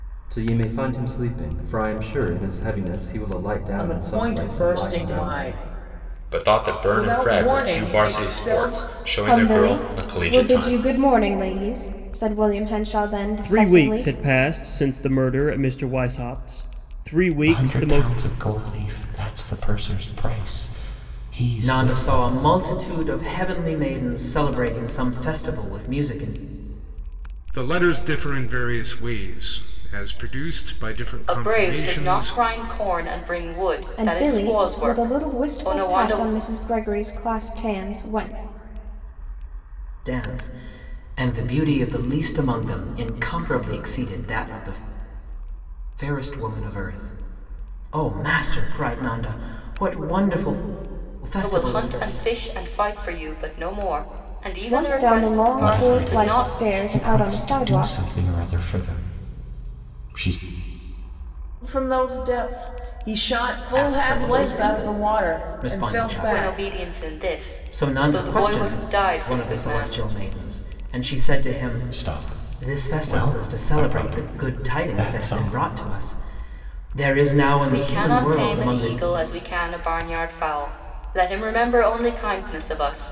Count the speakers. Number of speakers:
9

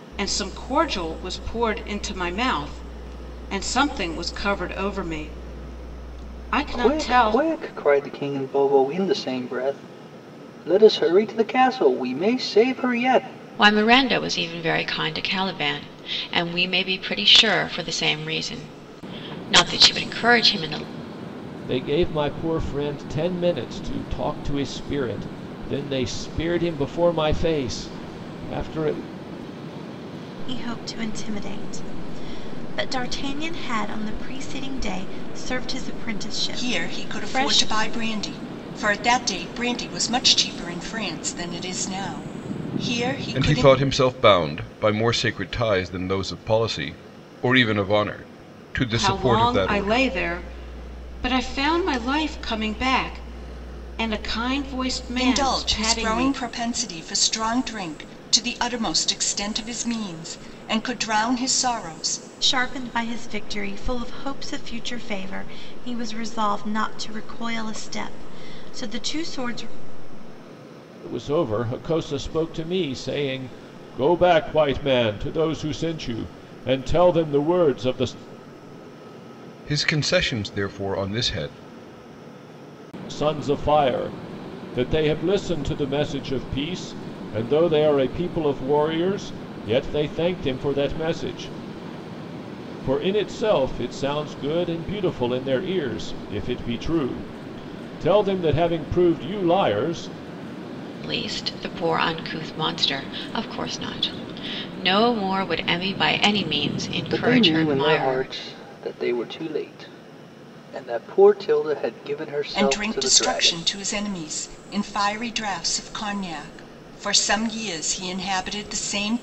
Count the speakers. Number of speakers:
7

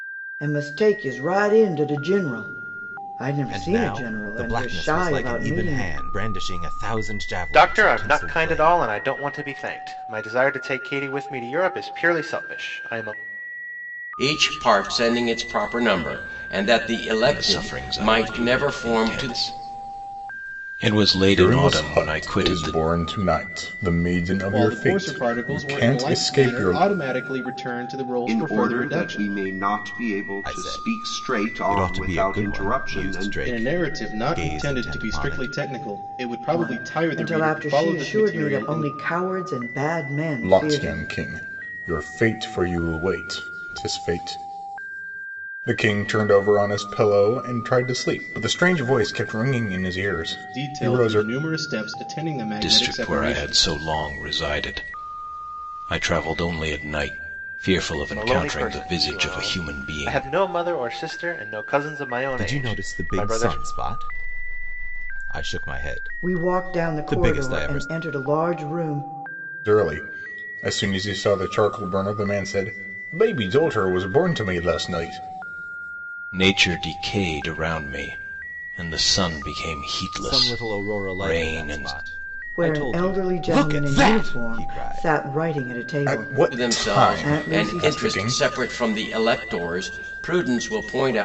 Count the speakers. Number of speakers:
8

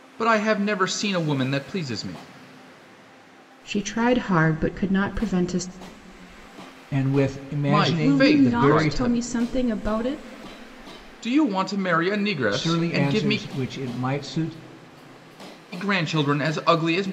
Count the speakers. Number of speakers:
3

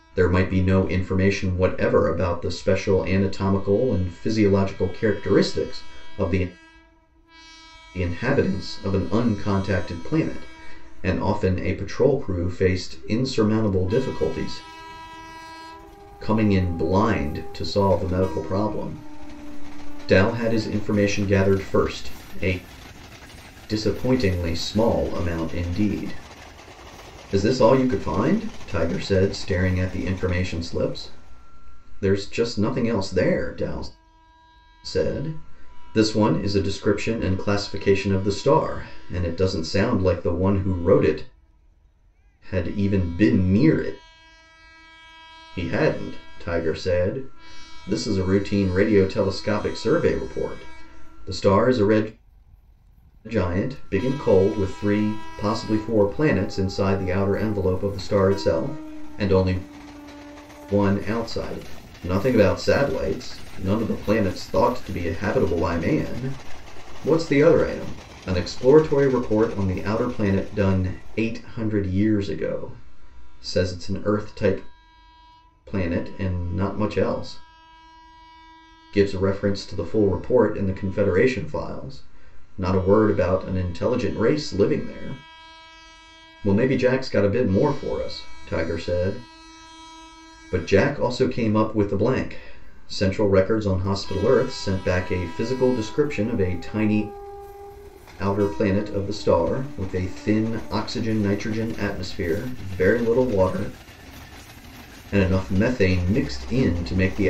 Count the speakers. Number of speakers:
1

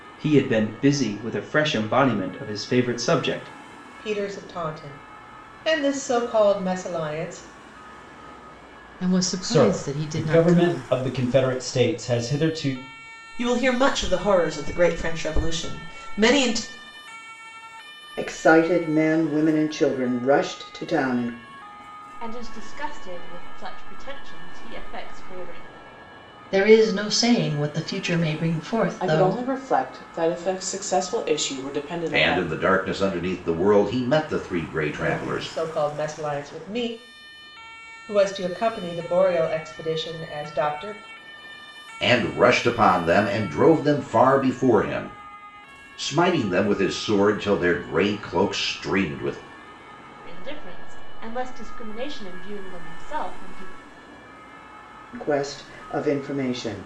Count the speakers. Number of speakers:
10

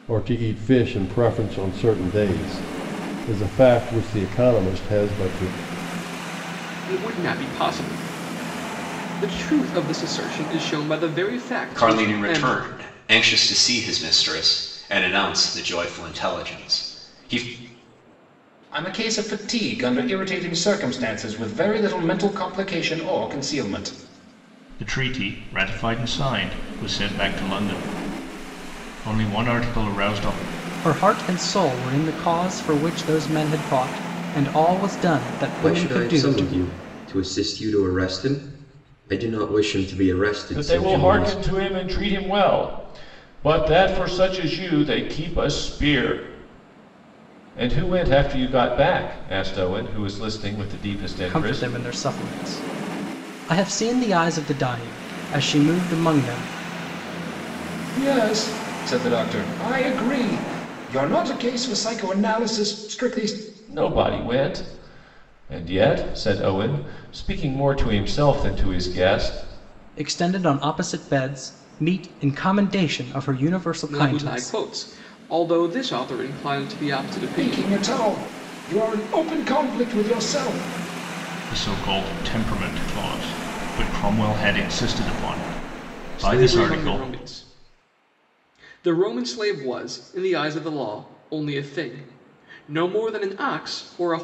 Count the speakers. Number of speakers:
8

